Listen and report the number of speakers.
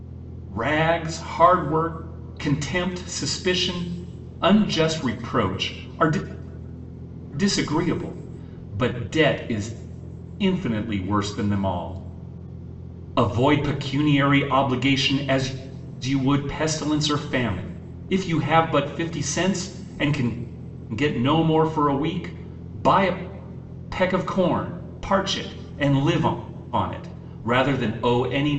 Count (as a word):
one